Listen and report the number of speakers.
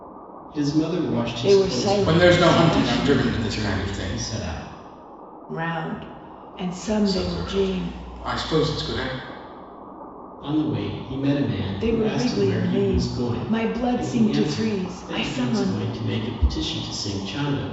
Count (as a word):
three